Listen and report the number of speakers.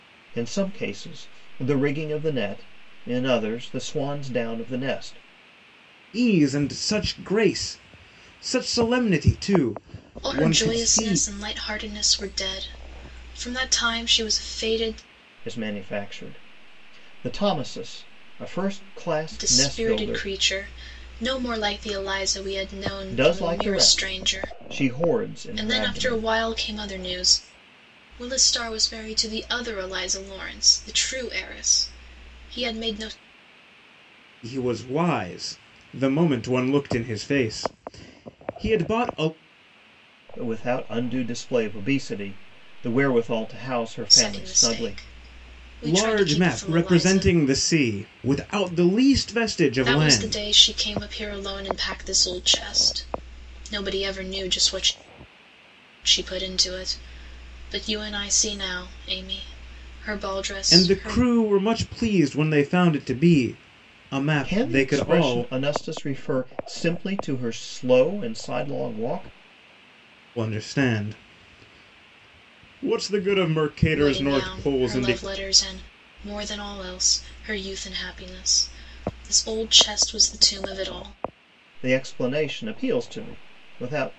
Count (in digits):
3